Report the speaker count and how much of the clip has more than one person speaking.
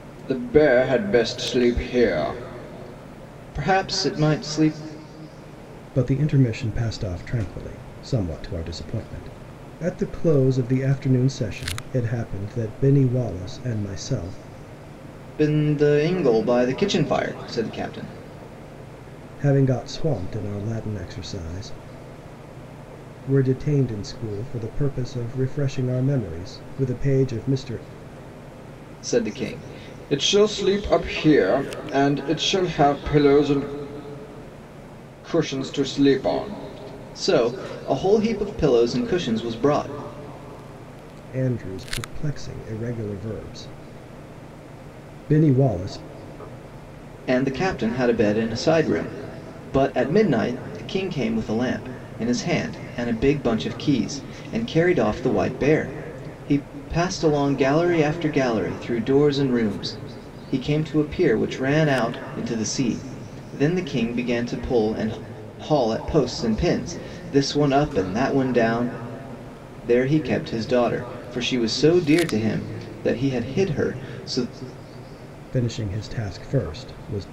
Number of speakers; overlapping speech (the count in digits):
2, no overlap